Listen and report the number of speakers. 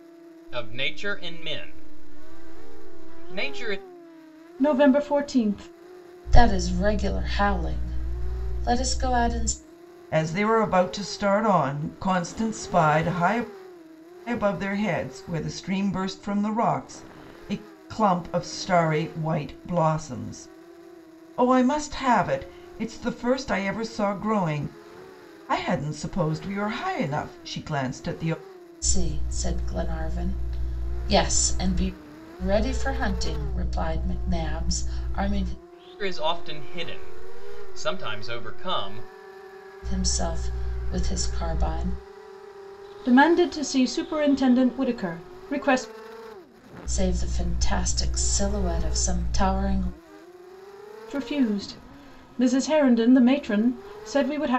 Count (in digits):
4